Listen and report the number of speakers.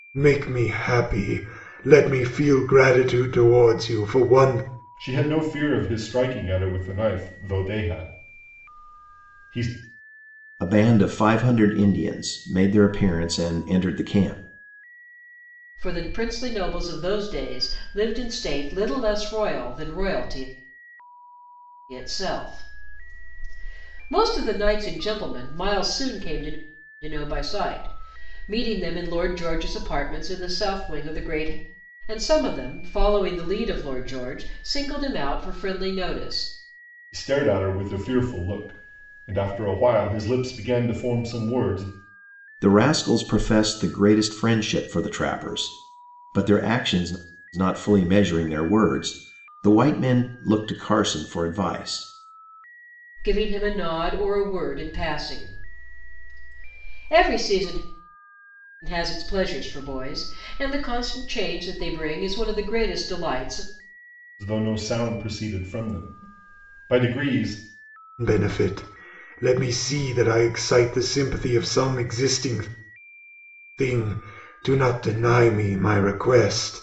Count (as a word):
four